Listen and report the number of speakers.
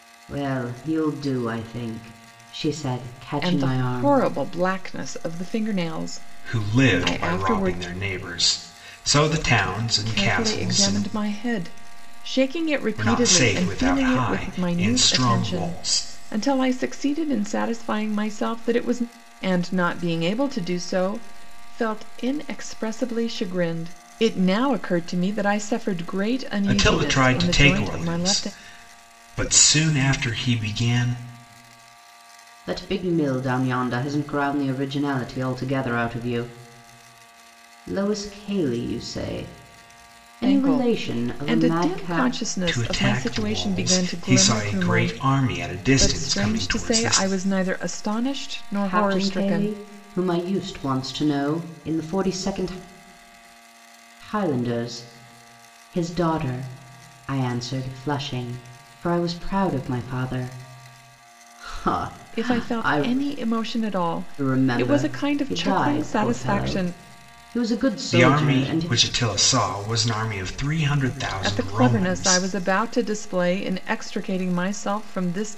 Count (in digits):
3